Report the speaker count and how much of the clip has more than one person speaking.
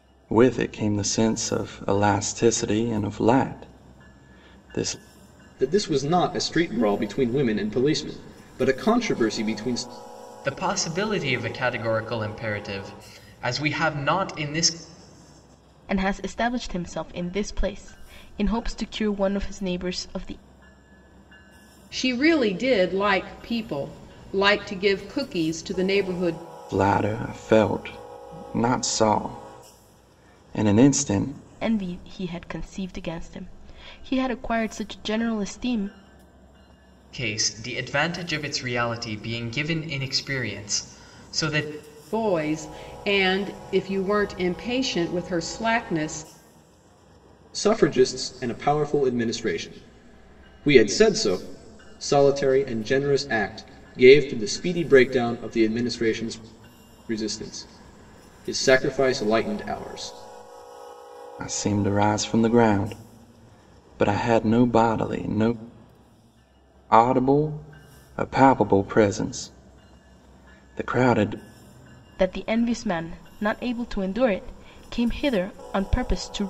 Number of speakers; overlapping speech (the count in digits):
5, no overlap